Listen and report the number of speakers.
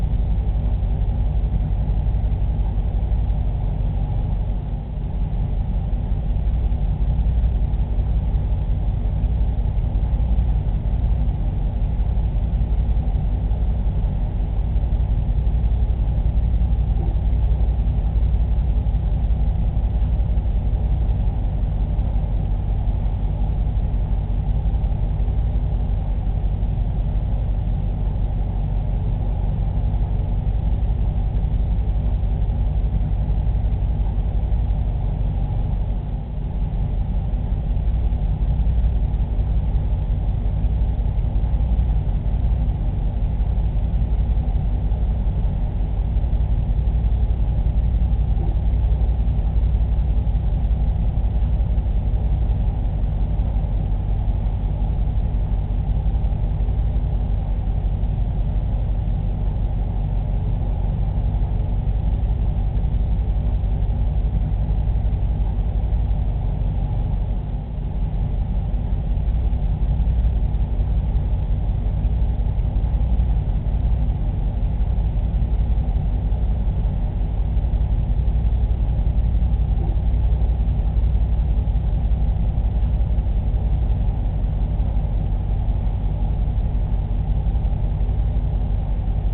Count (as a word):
zero